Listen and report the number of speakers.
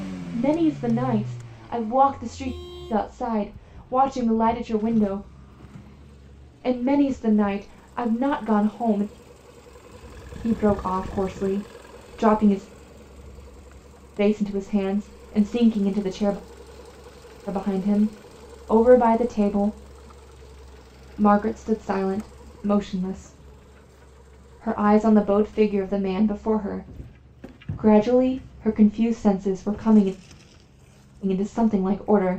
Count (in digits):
1